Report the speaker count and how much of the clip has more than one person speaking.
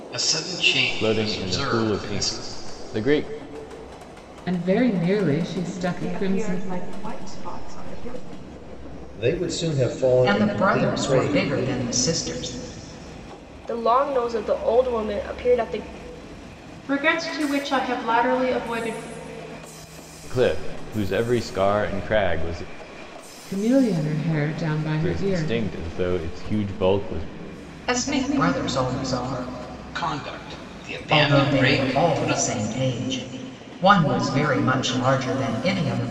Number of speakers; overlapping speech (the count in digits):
8, about 15%